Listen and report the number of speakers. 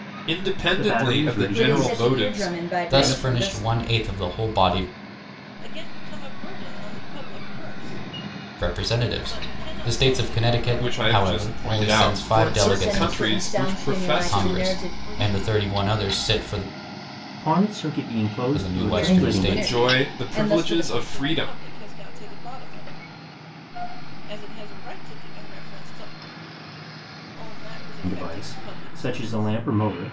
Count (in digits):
5